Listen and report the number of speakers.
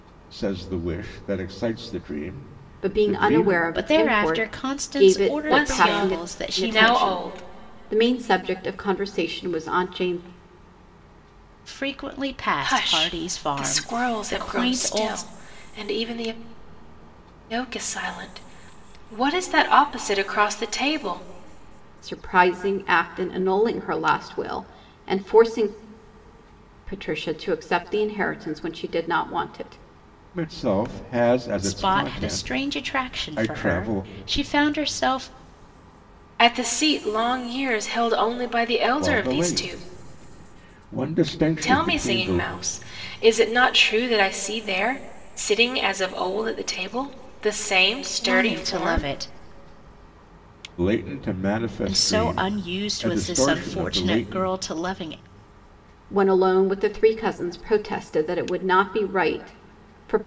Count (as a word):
four